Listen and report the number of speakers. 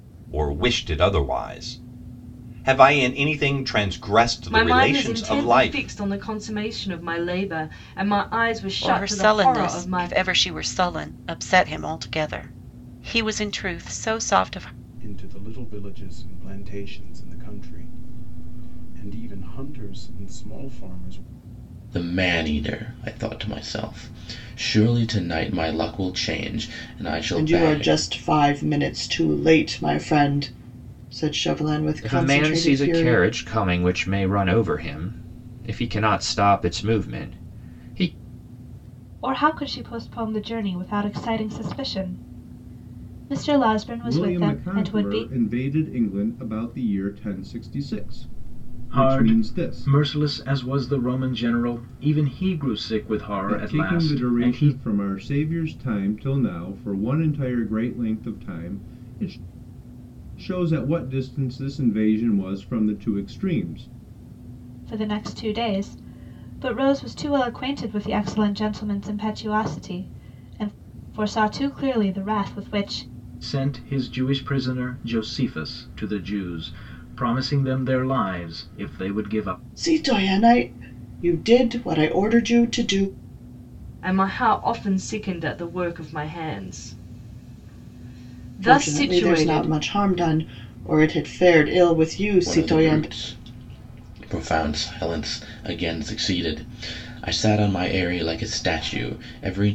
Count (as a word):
ten